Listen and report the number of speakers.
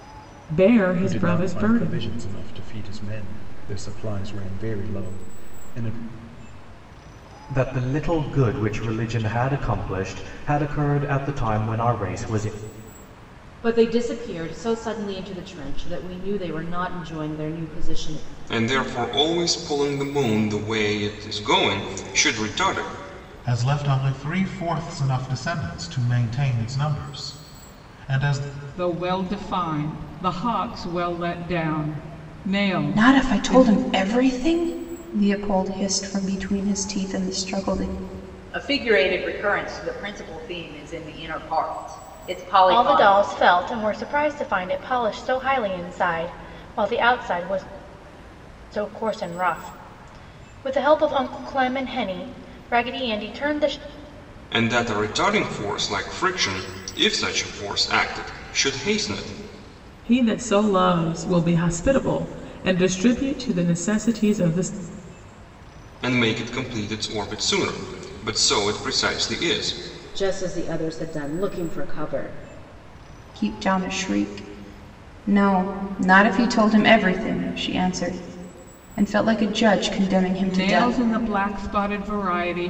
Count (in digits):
10